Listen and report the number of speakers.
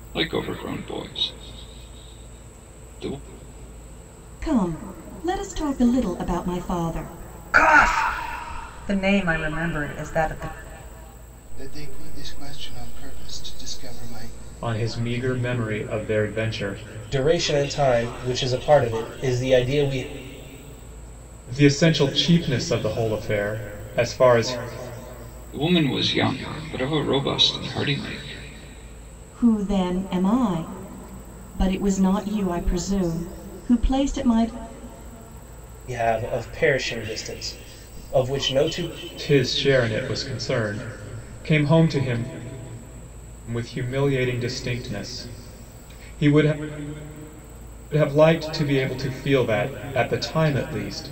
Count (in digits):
6